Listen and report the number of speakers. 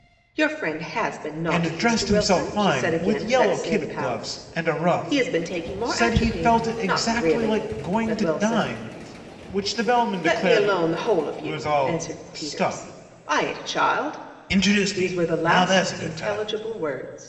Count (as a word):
two